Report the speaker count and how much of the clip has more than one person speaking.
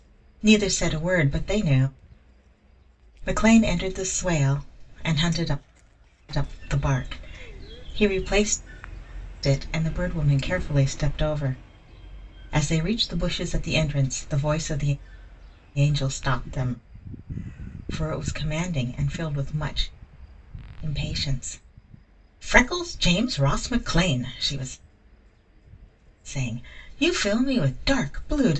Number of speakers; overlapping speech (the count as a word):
one, no overlap